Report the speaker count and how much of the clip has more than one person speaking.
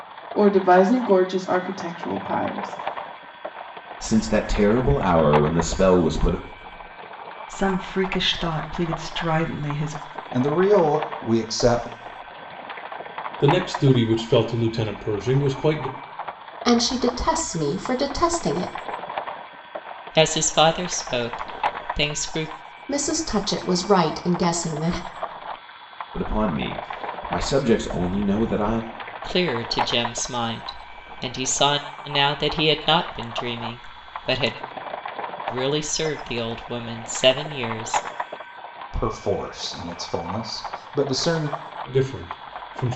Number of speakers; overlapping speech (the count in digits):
7, no overlap